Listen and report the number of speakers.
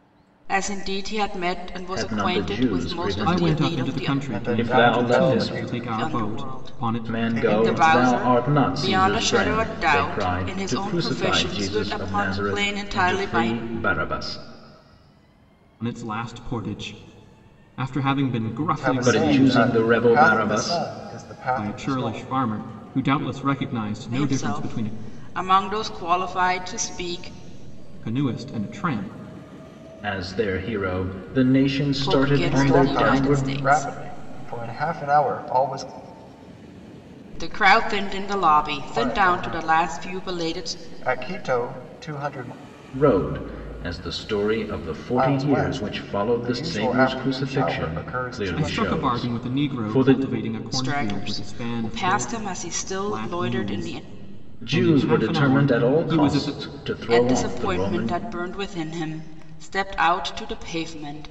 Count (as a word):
four